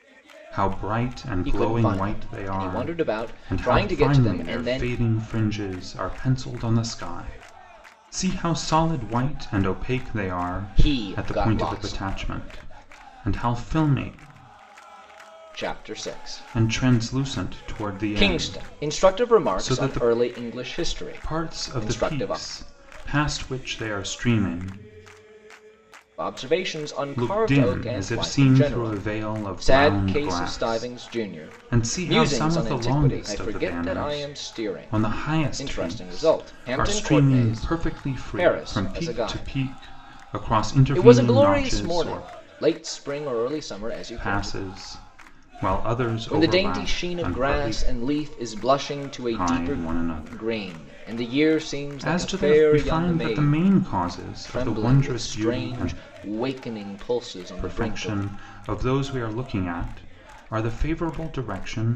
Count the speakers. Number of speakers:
2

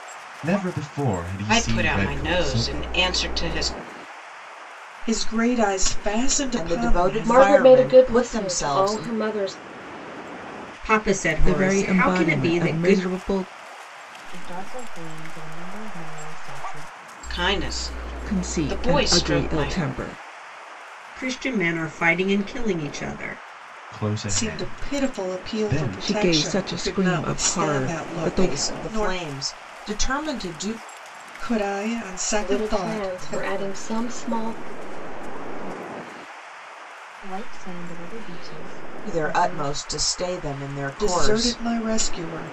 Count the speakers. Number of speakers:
8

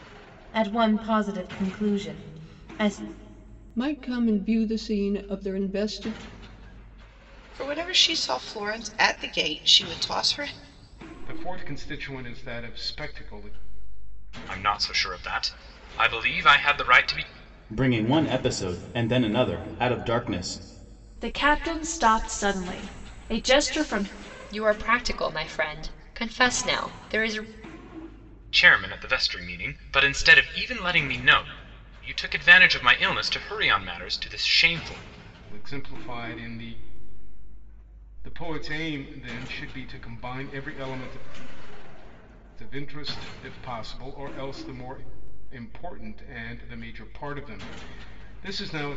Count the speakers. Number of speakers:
8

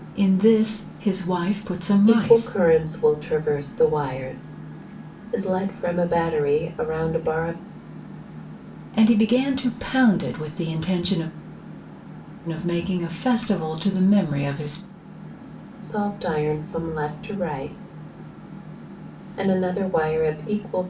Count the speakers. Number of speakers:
2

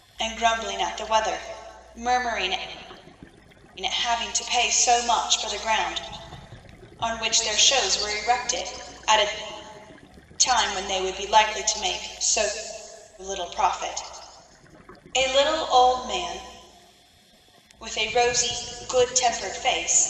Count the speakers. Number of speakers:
1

